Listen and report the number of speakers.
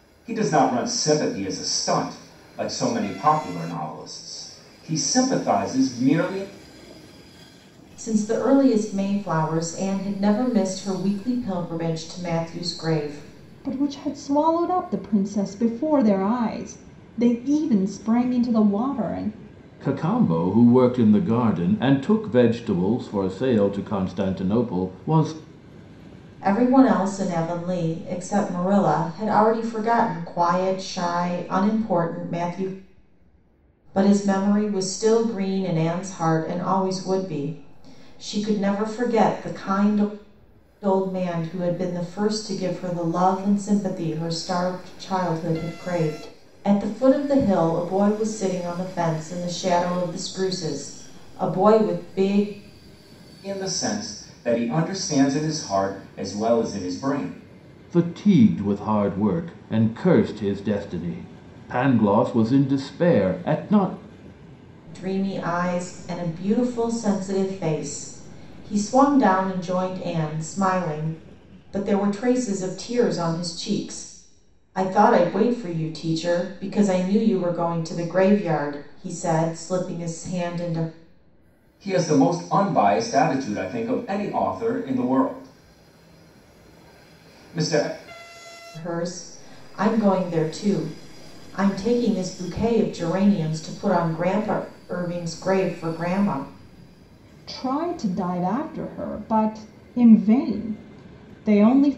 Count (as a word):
four